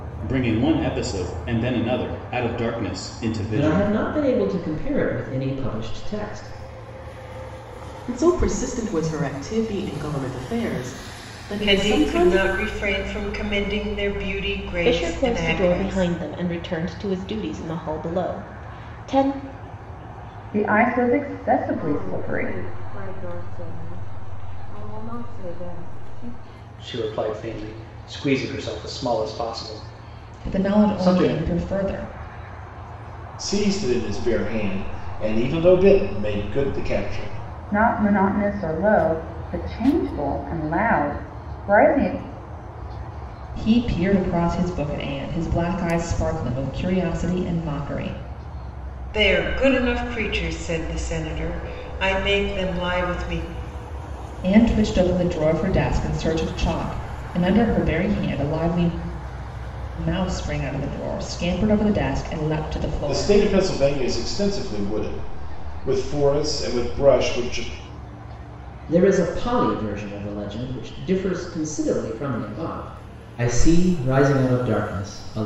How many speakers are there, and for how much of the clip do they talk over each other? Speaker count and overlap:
10, about 6%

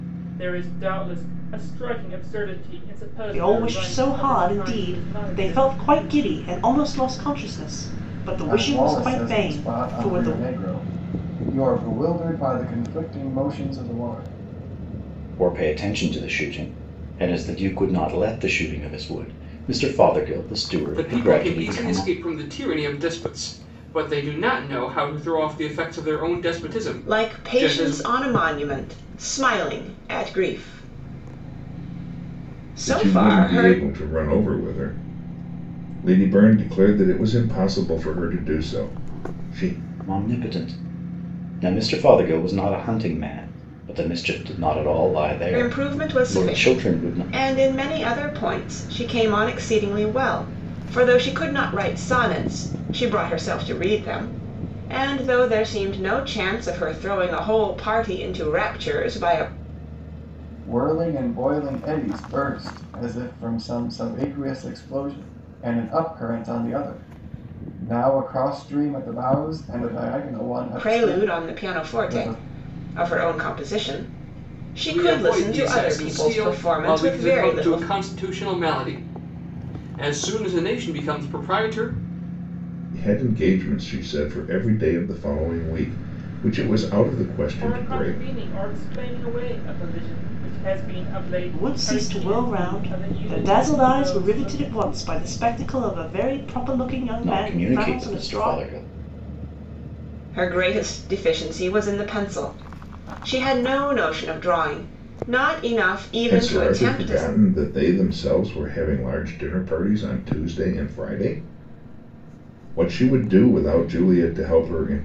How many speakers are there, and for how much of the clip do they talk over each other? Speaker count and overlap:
7, about 18%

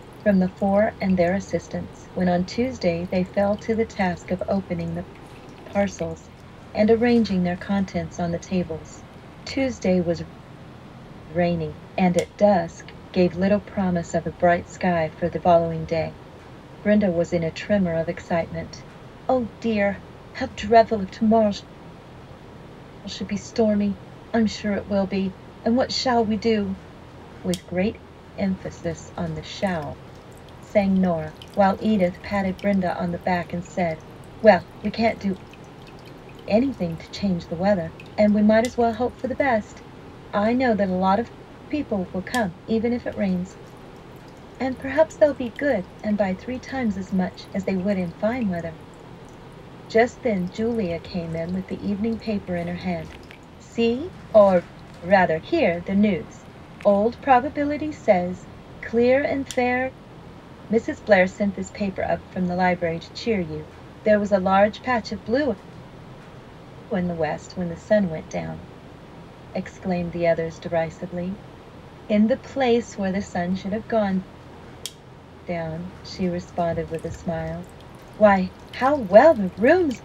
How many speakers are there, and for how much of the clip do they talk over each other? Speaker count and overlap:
1, no overlap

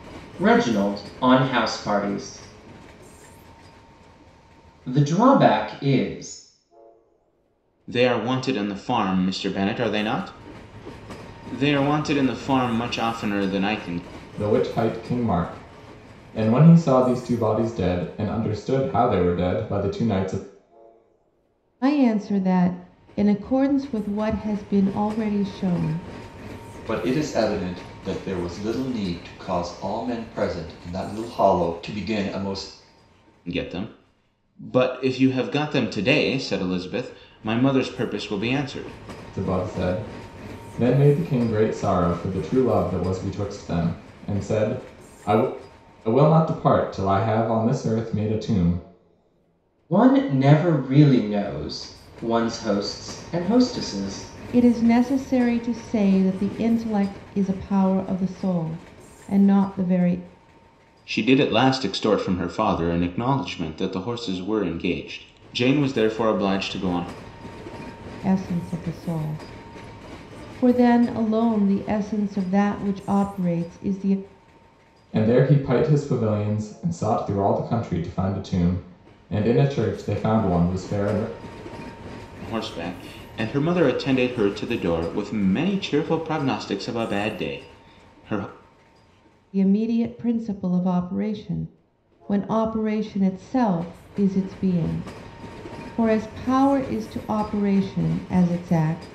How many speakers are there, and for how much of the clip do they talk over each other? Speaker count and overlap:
5, no overlap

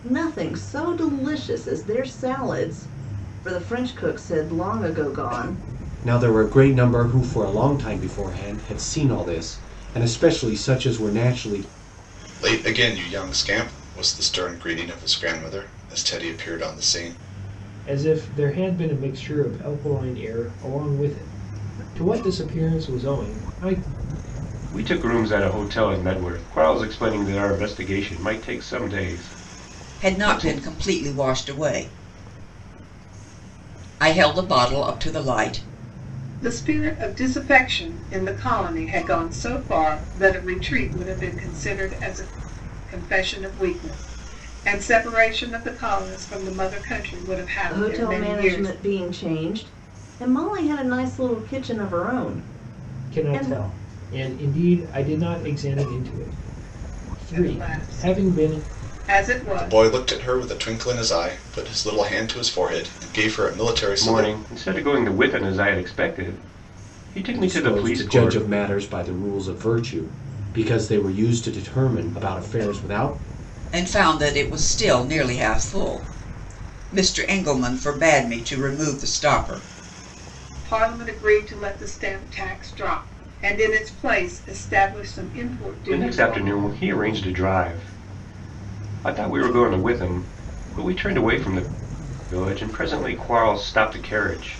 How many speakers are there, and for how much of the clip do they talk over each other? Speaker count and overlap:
7, about 7%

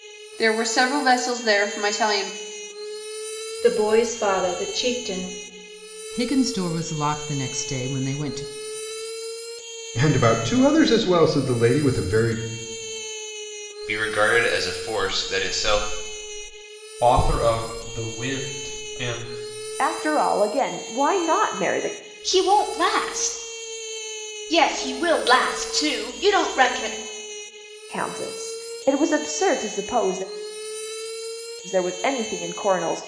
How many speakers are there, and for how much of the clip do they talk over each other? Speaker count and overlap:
8, no overlap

